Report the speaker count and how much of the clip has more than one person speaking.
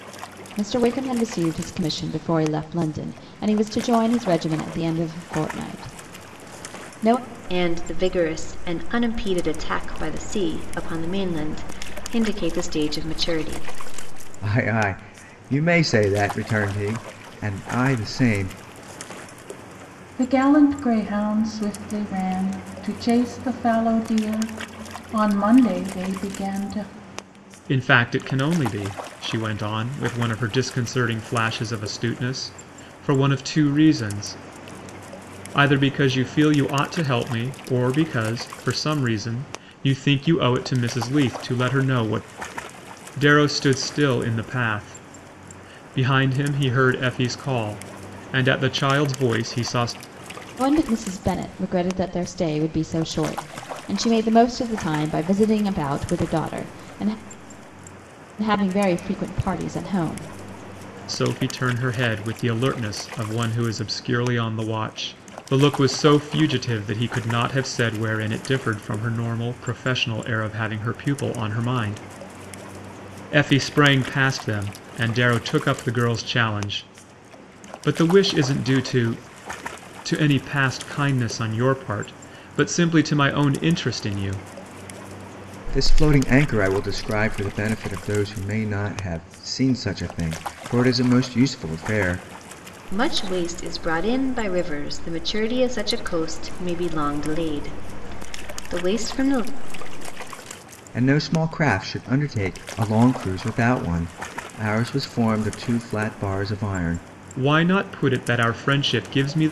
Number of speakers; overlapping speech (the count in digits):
5, no overlap